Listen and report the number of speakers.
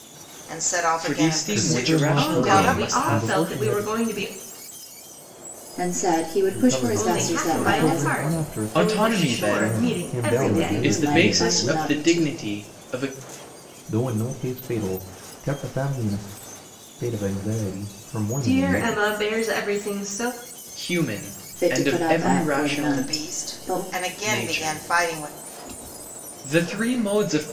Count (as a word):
five